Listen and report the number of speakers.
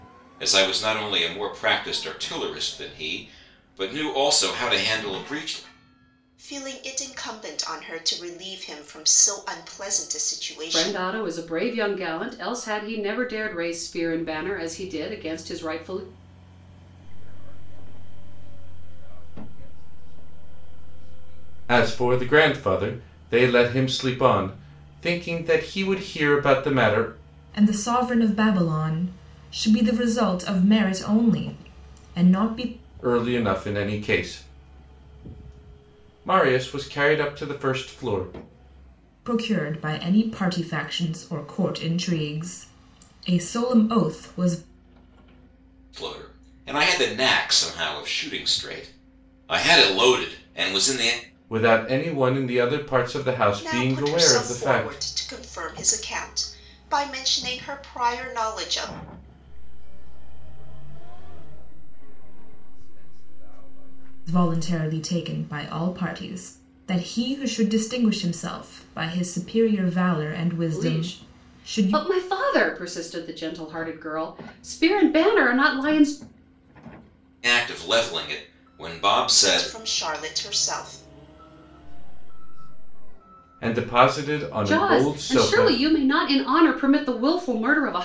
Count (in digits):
6